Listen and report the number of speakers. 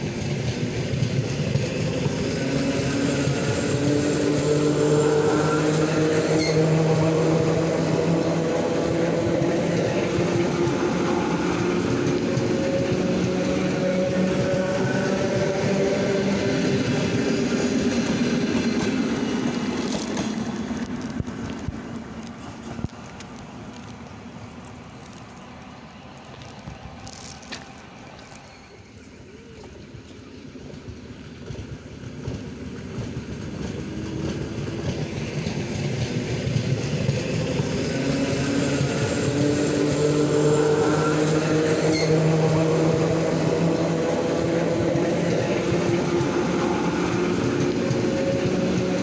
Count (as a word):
zero